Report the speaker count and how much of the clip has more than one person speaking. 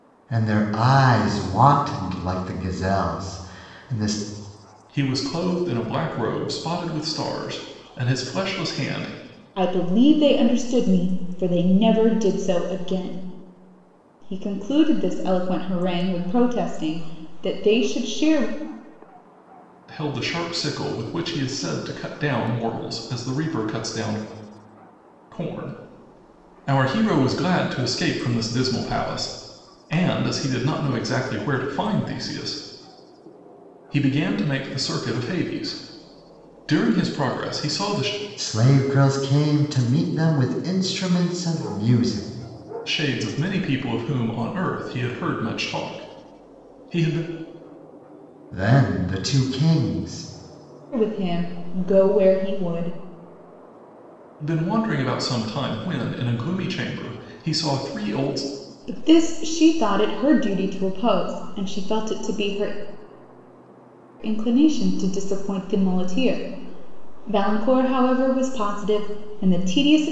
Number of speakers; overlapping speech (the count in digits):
3, no overlap